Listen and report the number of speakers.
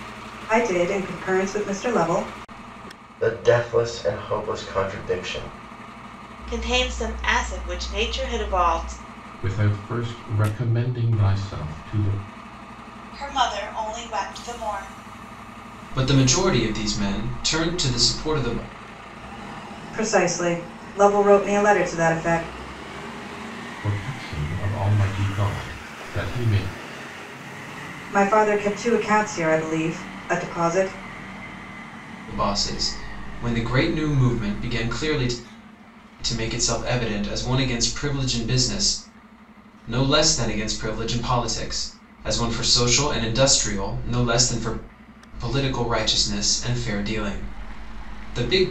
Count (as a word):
six